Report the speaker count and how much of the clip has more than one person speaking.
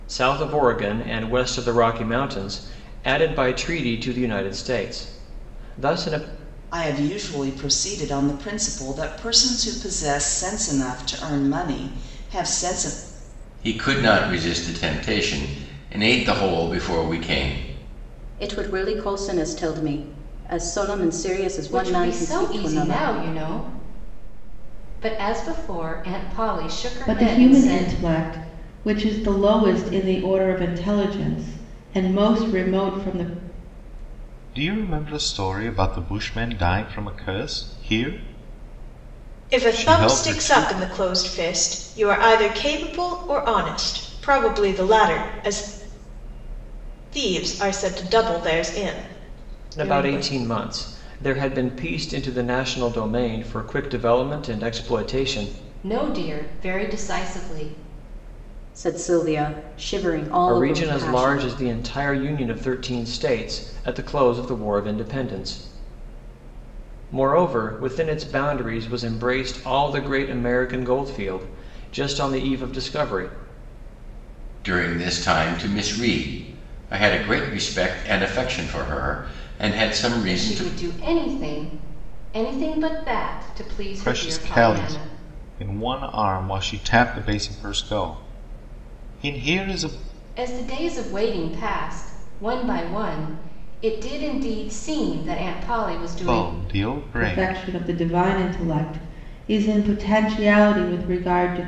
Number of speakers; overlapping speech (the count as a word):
eight, about 8%